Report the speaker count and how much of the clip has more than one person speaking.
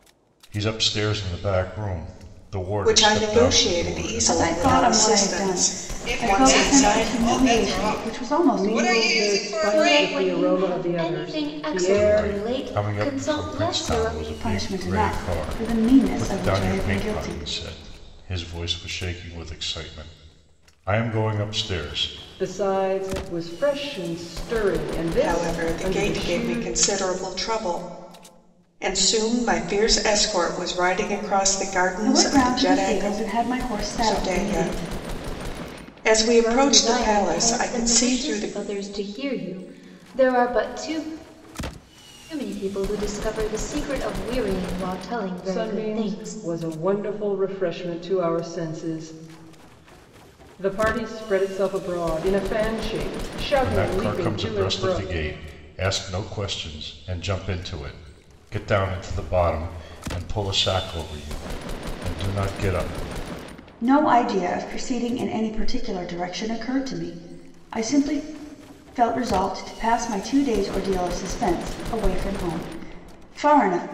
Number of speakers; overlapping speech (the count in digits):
6, about 31%